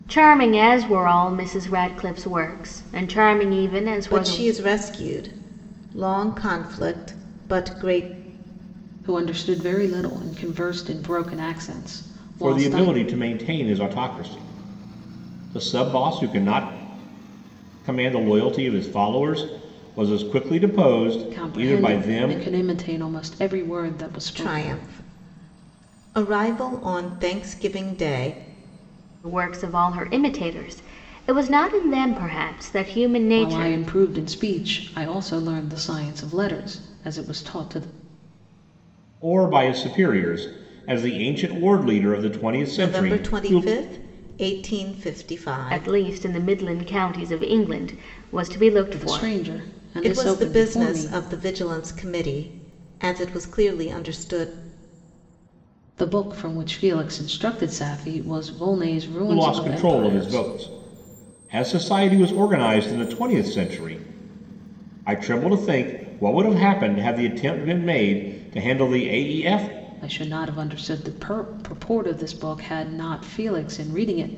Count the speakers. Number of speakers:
four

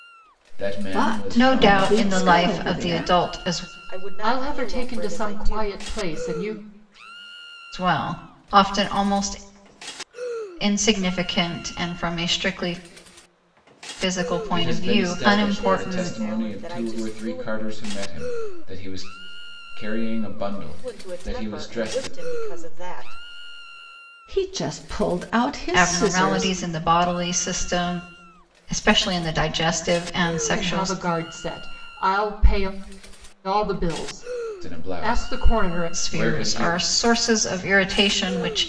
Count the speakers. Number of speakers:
five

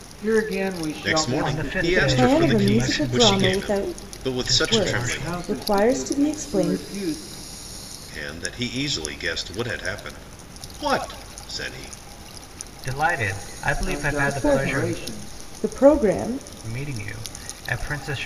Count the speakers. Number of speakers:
four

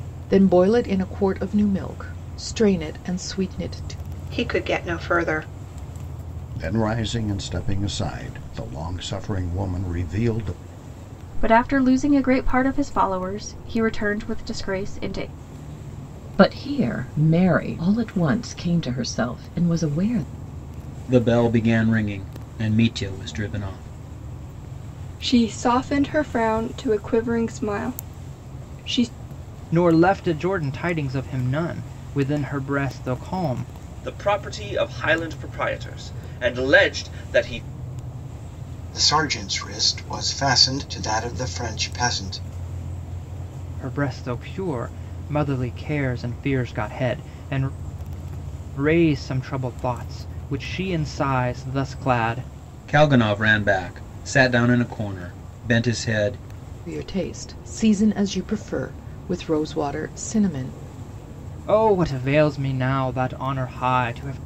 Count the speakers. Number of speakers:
ten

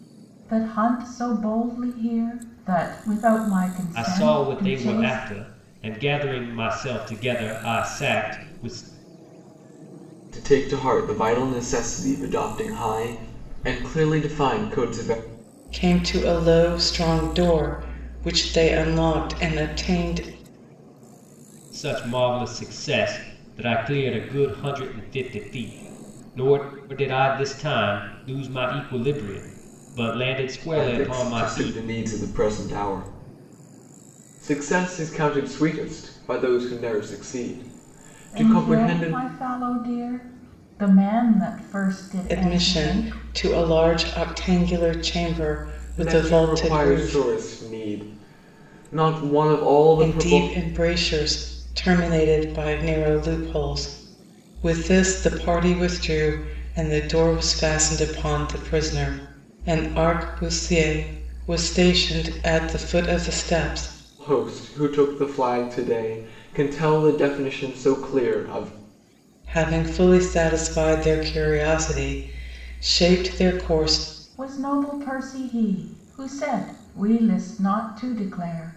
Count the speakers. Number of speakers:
four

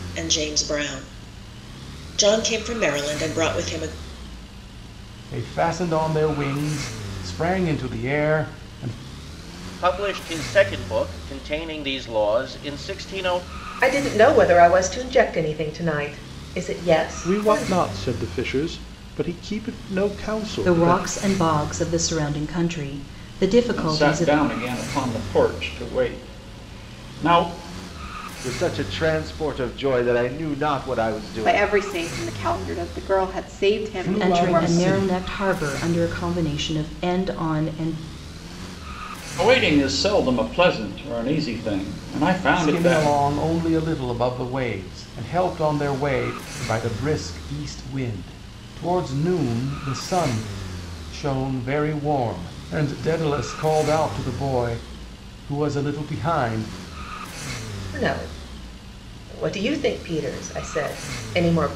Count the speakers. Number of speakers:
nine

